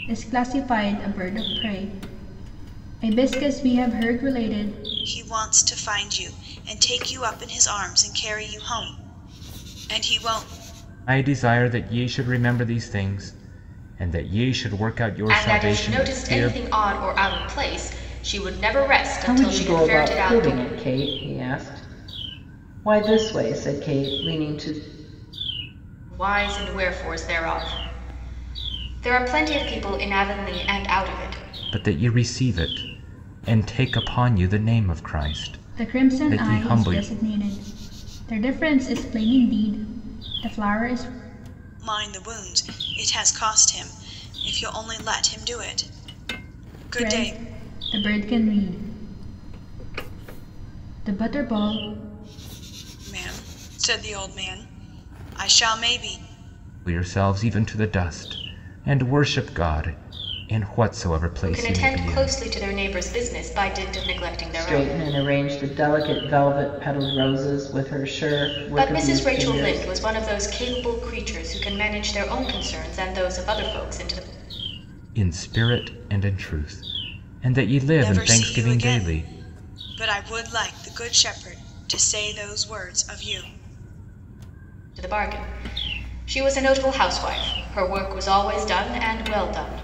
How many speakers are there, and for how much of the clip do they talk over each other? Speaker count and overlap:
5, about 10%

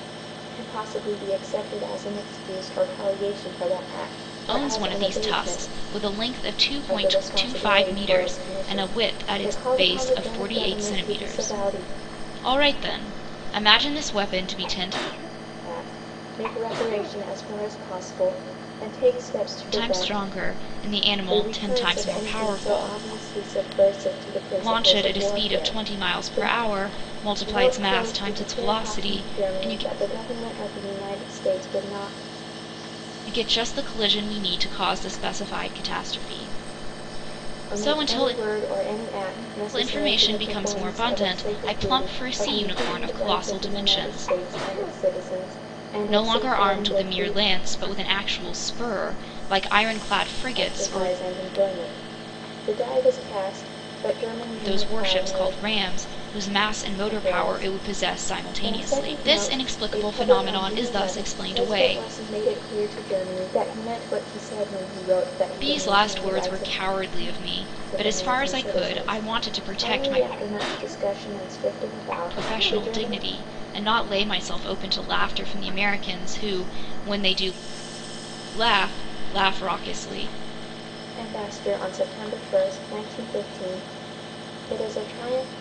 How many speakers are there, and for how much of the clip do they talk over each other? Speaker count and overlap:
2, about 36%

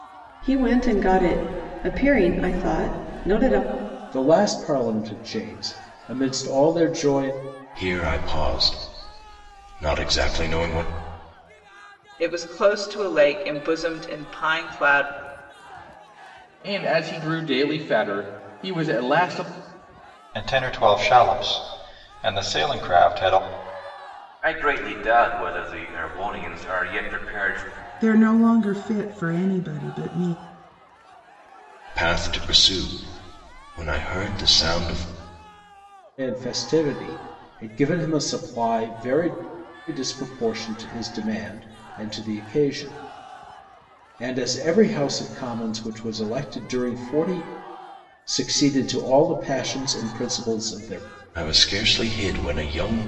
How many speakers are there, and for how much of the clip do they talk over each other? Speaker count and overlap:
8, no overlap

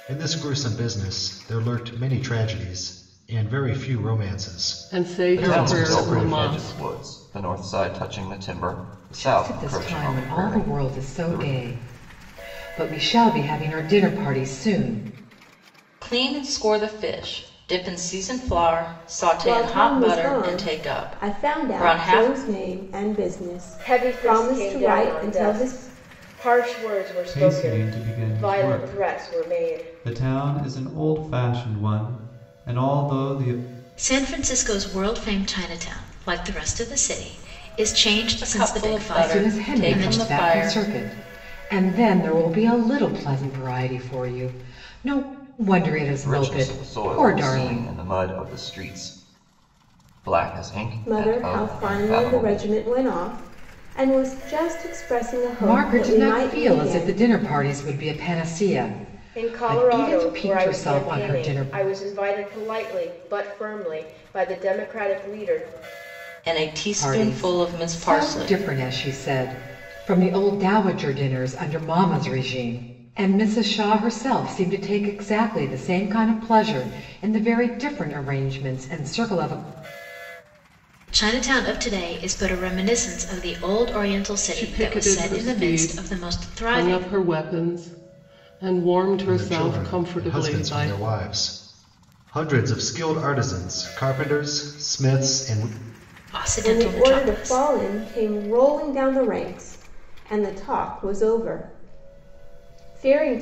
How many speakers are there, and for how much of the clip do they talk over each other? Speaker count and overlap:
9, about 28%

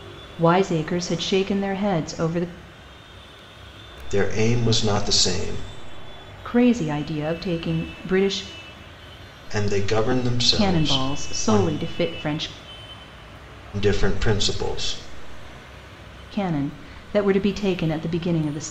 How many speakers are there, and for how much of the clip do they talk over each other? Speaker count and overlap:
2, about 7%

